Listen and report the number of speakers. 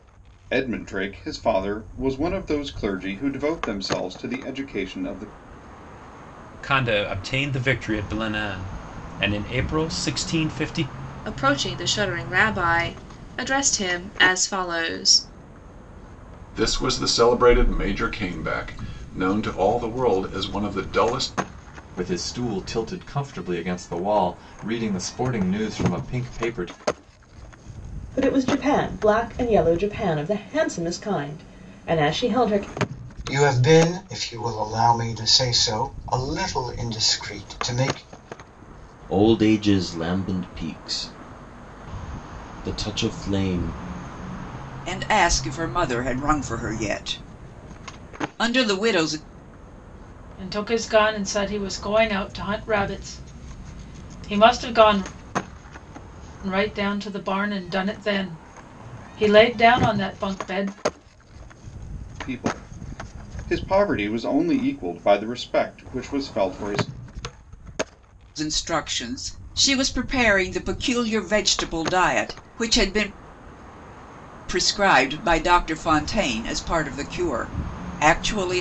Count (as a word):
ten